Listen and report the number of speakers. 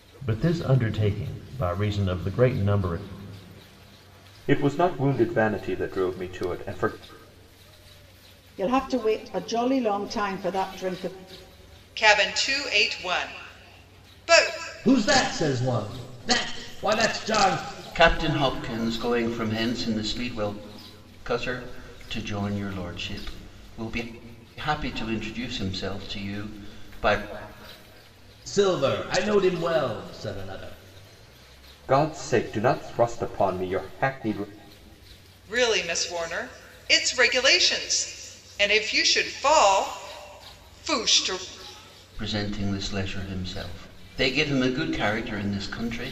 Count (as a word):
six